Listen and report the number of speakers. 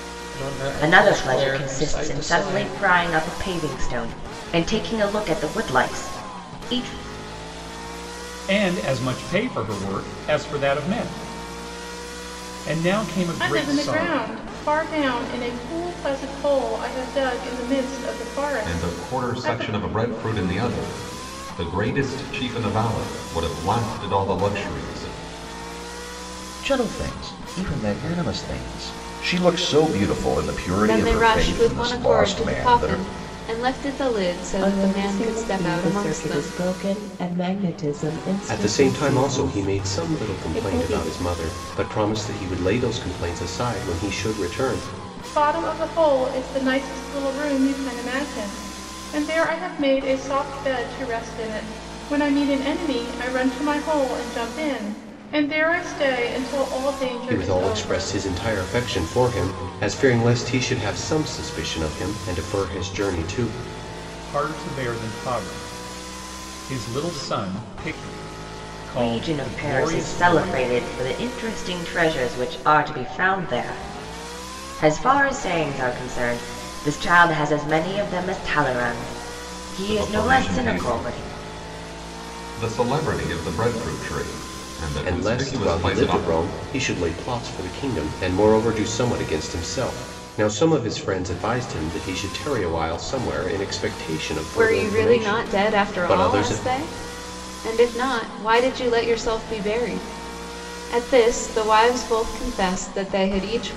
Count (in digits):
9